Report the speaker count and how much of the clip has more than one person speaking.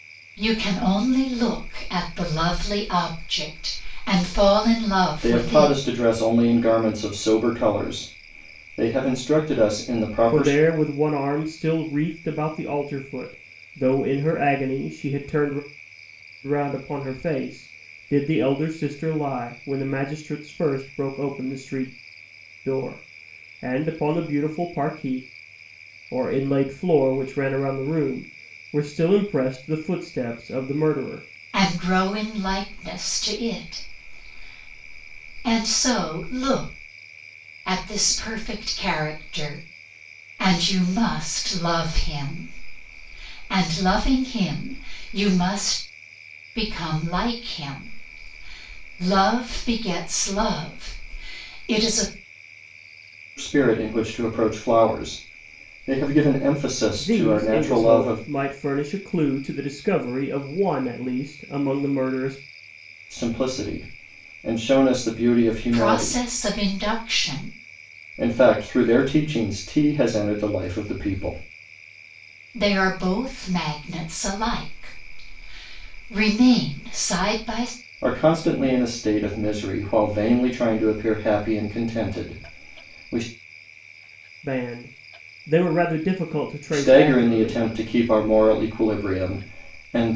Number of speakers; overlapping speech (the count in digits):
3, about 4%